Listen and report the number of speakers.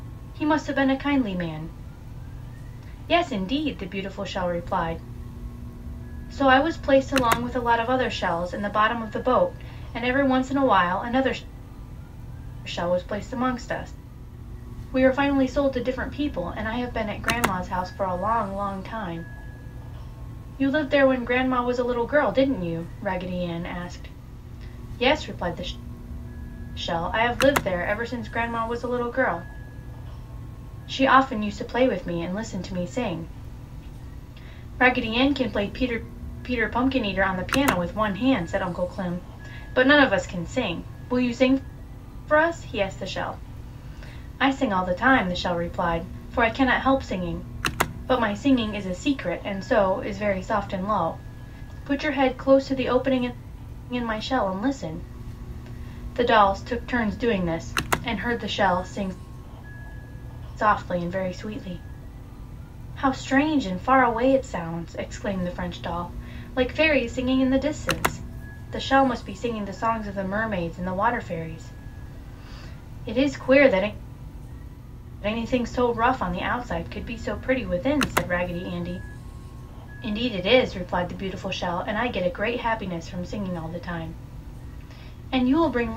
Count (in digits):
1